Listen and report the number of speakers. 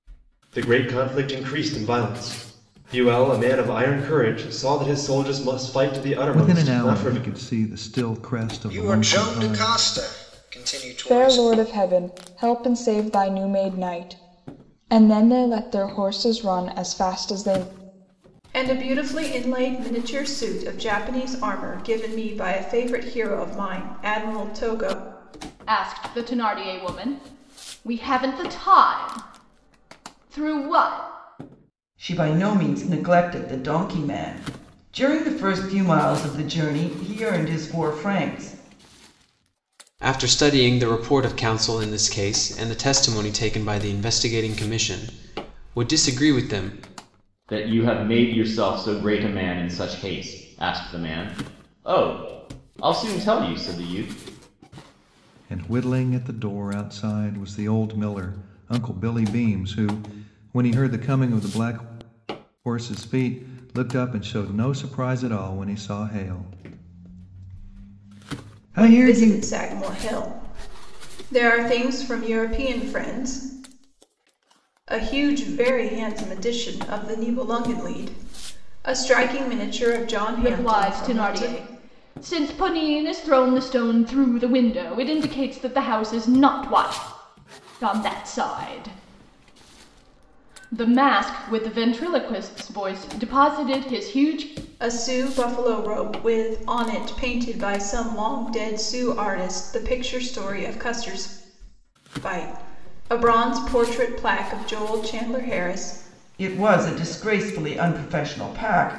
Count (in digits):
9